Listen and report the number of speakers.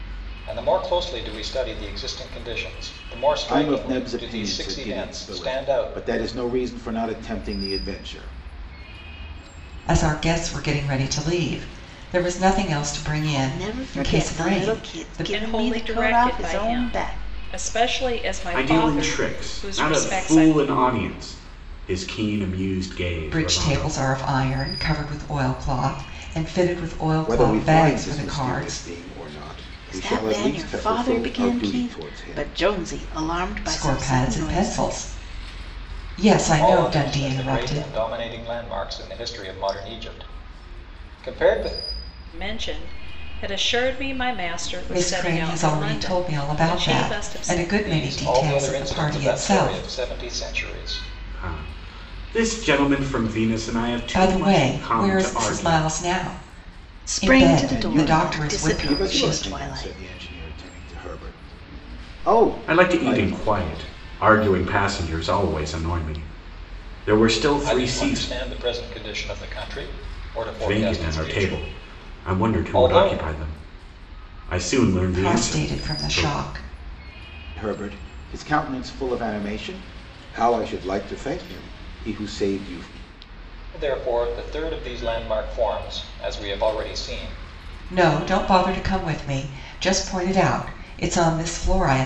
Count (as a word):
six